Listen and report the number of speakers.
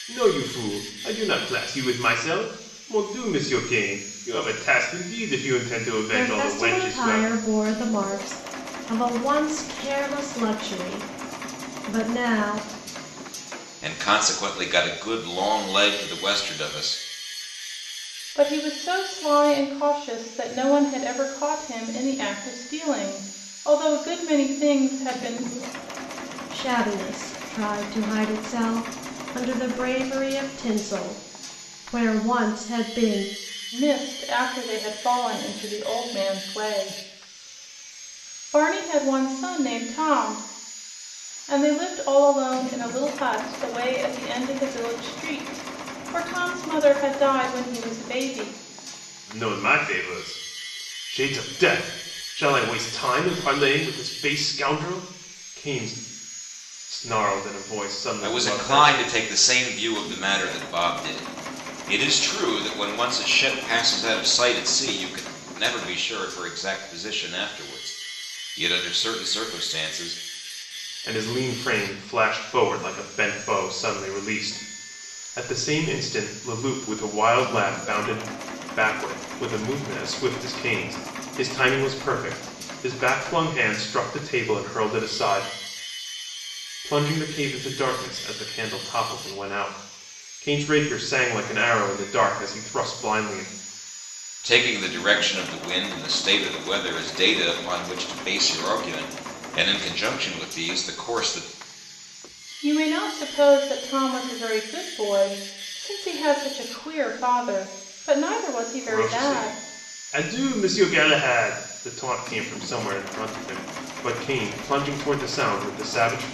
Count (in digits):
4